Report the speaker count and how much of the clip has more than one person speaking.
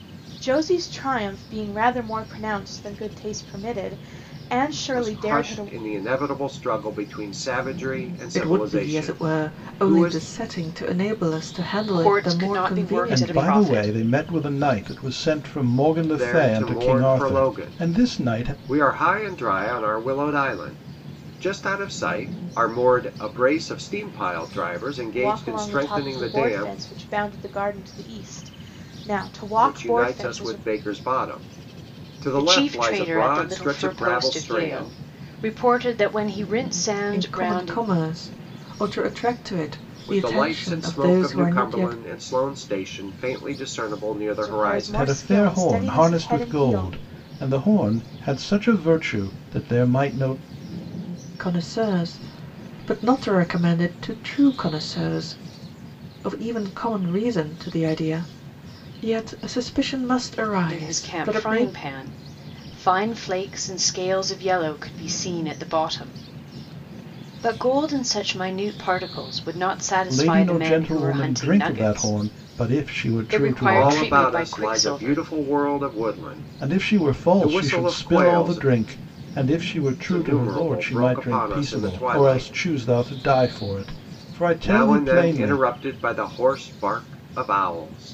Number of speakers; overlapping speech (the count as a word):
five, about 32%